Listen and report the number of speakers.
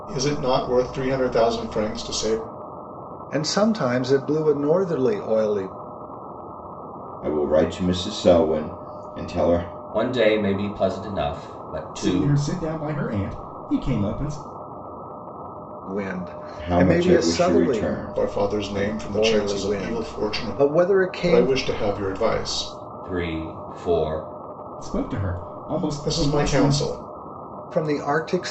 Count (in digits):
5